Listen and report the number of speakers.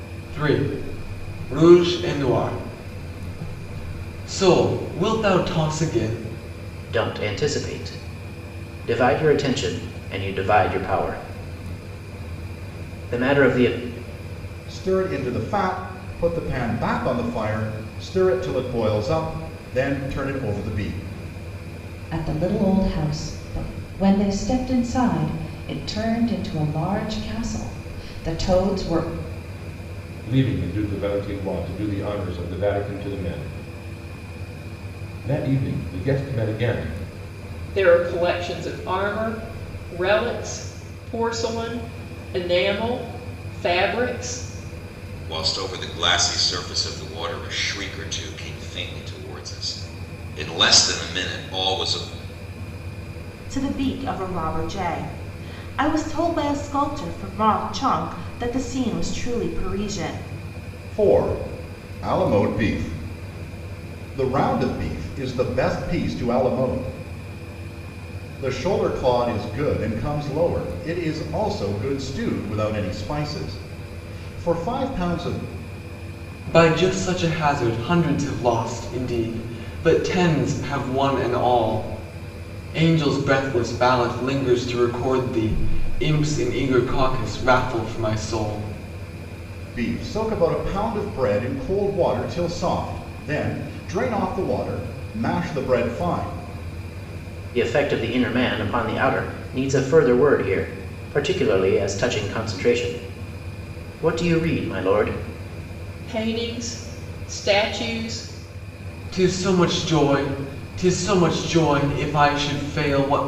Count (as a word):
eight